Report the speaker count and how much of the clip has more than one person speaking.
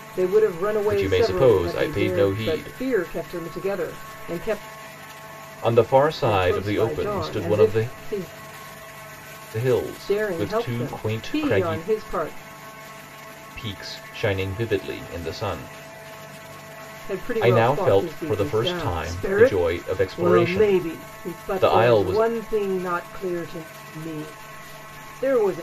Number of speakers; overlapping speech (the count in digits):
2, about 40%